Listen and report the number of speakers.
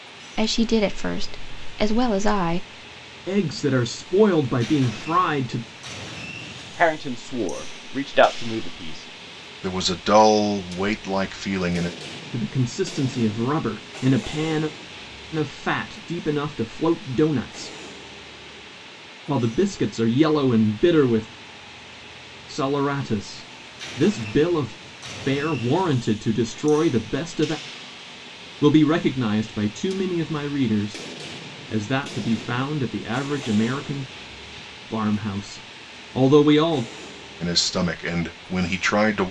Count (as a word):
four